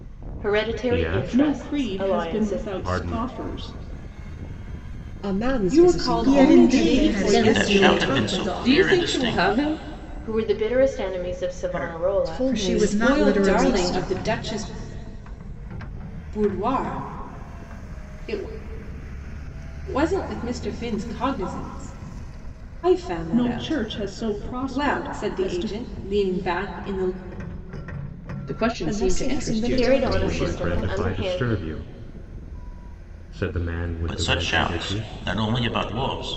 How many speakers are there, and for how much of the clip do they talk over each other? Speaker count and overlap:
9, about 42%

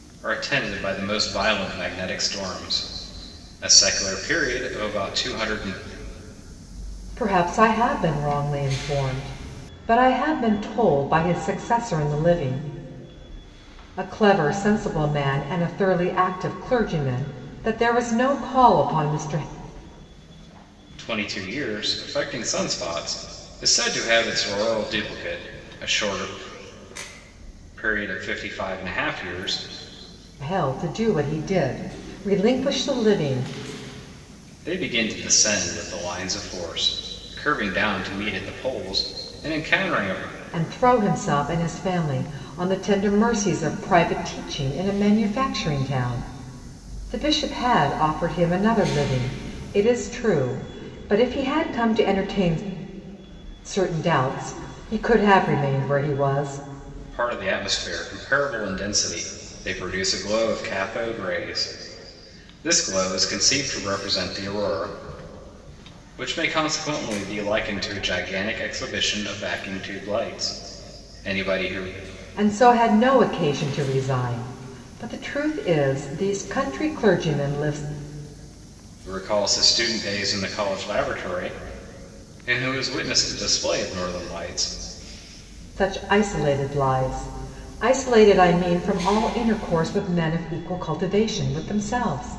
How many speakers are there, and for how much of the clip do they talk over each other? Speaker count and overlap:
2, no overlap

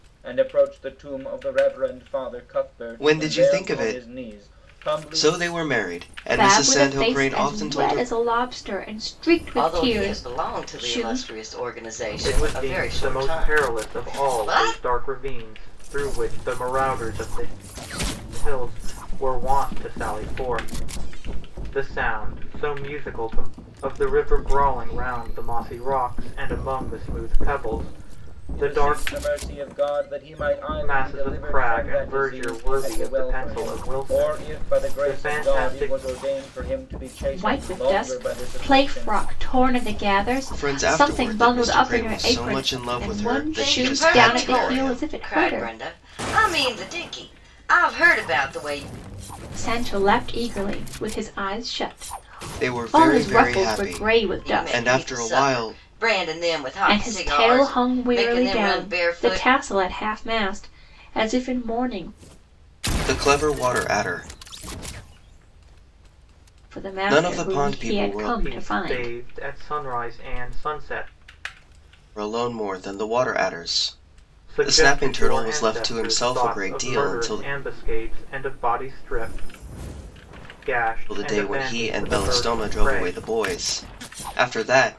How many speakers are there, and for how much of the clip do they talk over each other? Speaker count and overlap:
5, about 40%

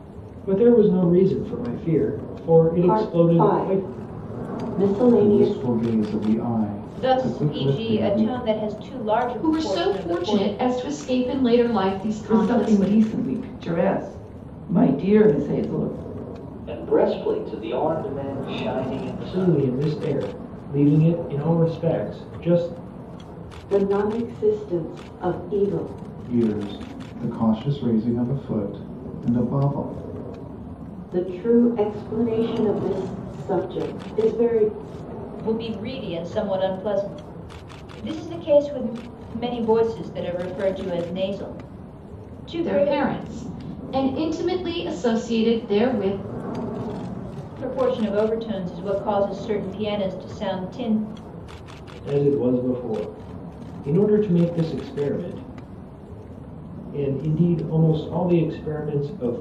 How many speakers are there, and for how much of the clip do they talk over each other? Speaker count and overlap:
7, about 10%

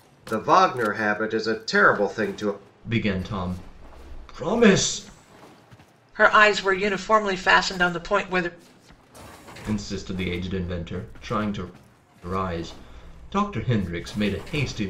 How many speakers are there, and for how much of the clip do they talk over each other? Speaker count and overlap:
3, no overlap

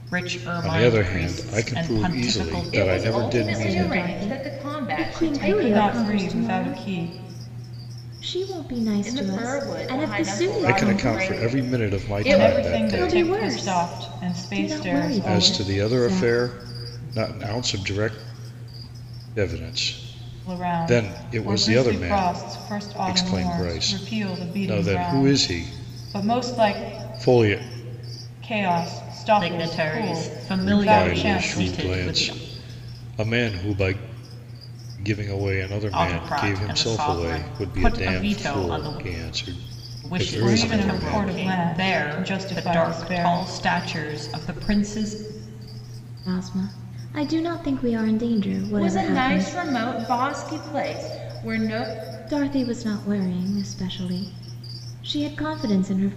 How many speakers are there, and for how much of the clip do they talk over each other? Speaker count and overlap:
5, about 52%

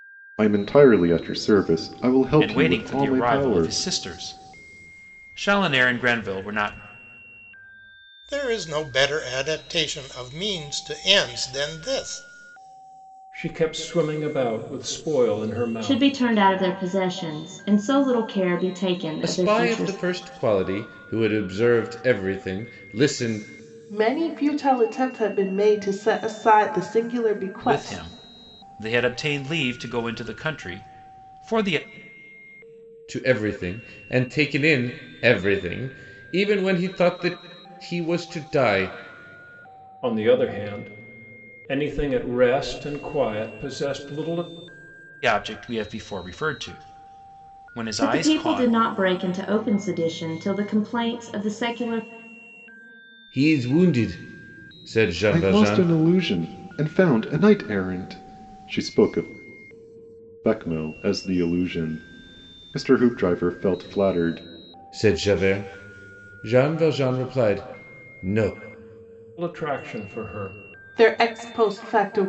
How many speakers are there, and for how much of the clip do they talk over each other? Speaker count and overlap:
7, about 6%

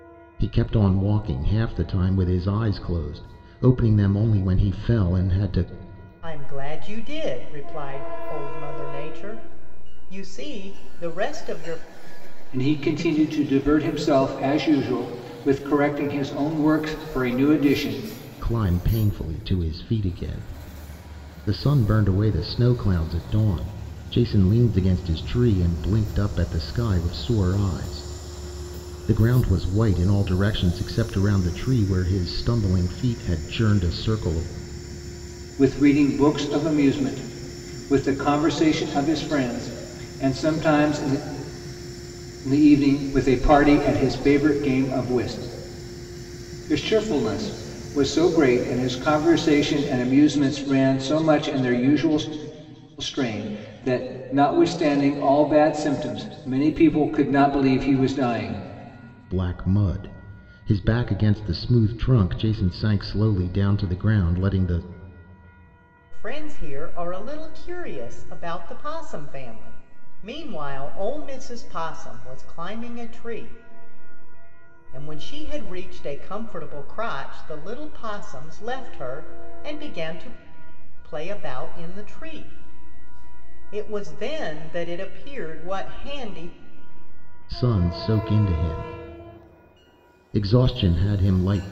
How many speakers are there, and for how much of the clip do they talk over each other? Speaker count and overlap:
3, no overlap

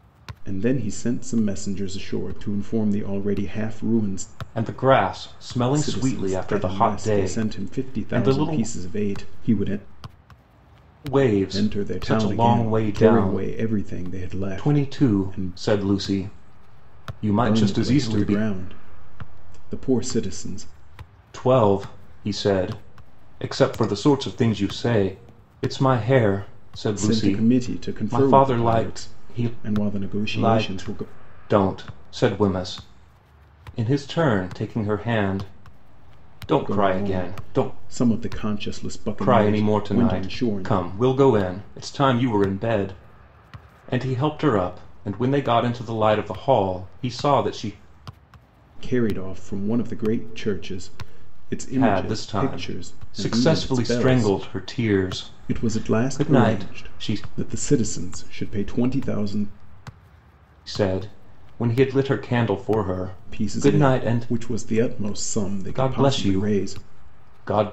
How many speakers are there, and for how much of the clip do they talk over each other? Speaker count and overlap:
2, about 28%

